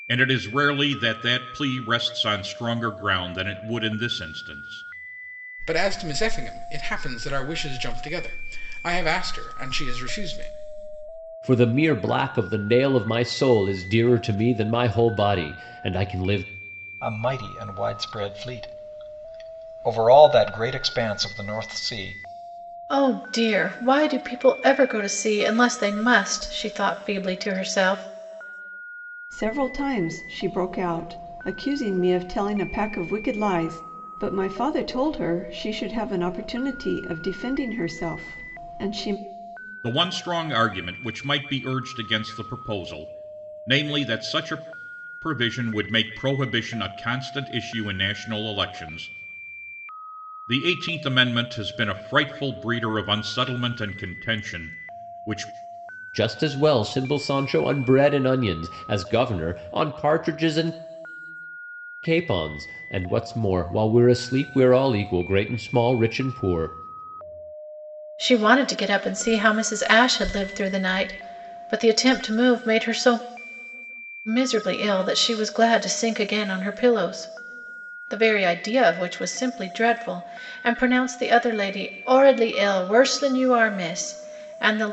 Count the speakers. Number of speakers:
six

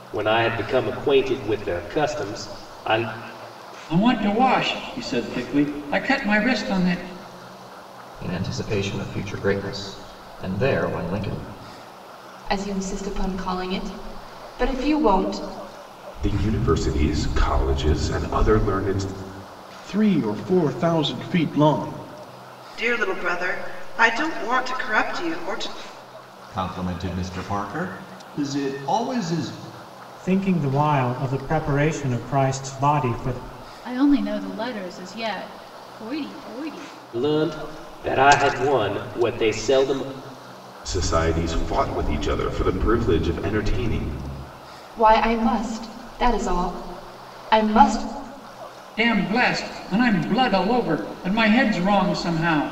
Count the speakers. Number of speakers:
ten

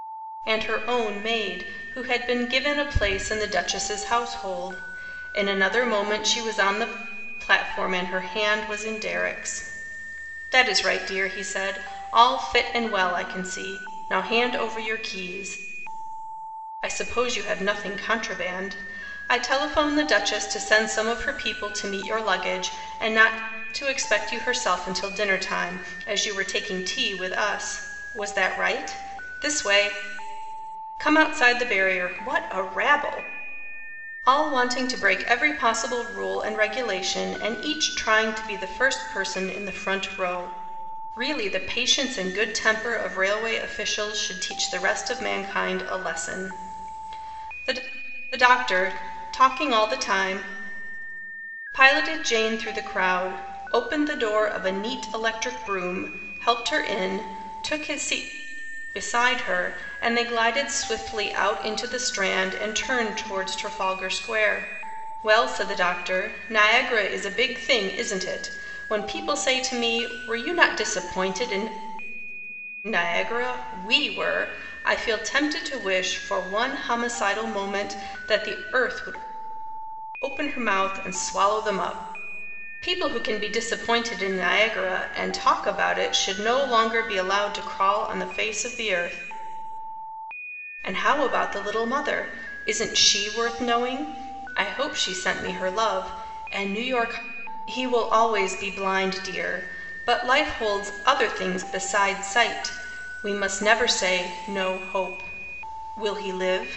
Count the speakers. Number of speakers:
one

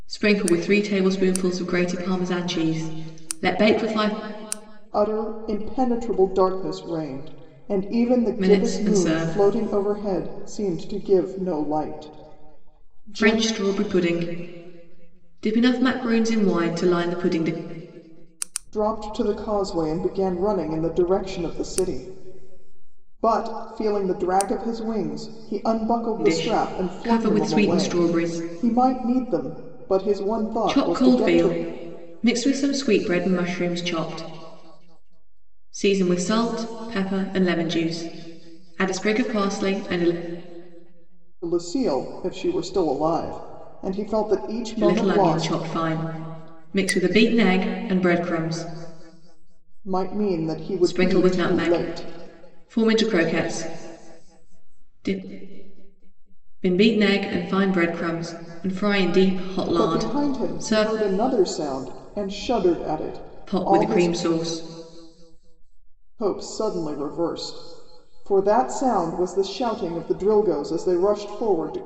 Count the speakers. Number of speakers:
two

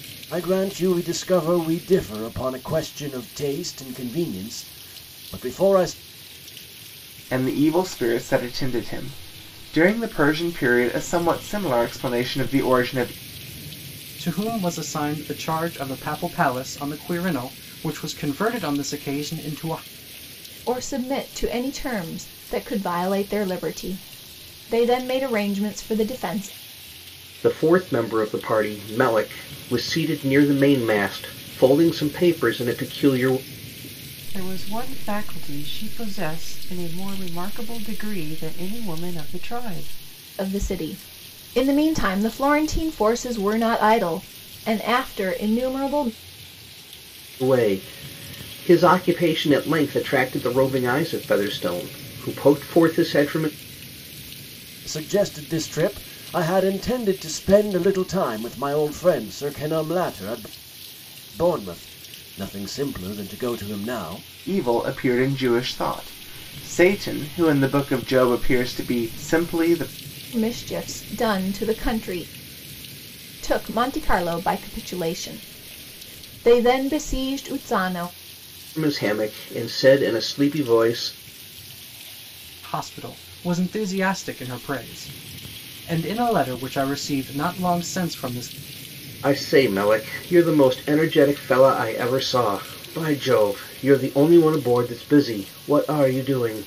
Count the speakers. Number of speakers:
six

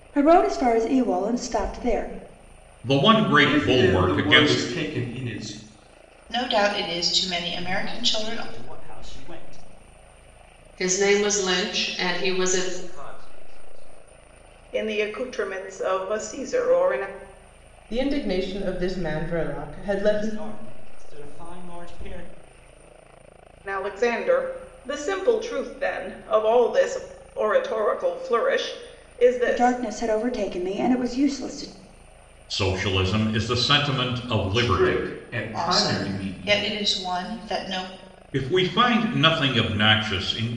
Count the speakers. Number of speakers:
nine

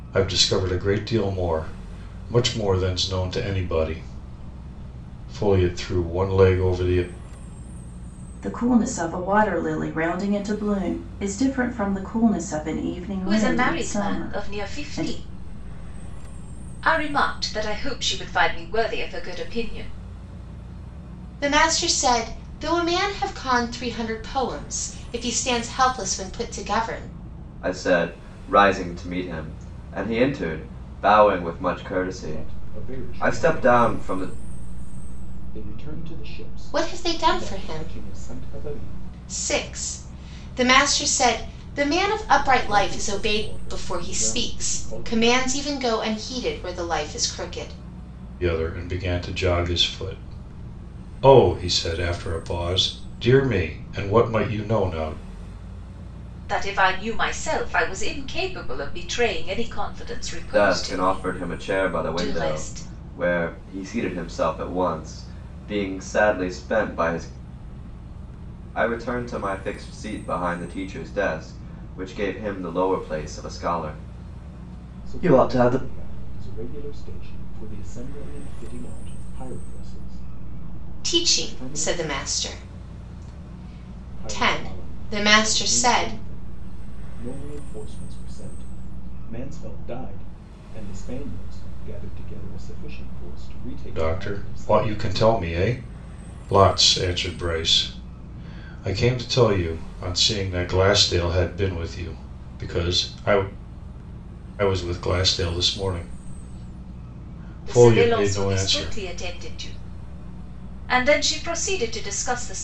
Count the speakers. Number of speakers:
six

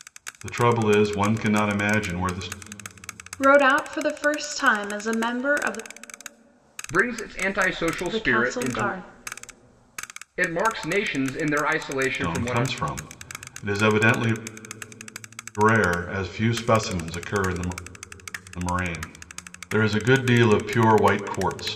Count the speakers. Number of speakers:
three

